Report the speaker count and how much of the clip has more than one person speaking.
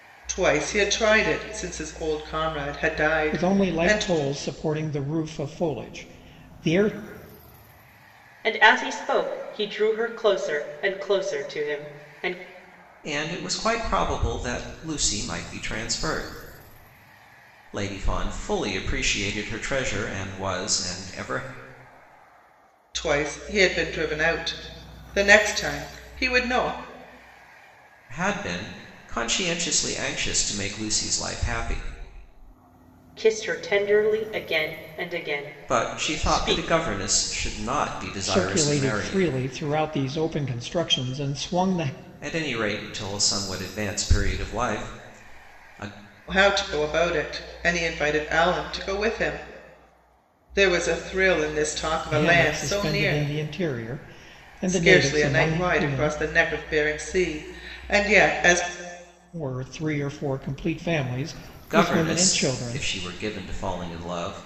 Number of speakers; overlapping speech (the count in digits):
4, about 11%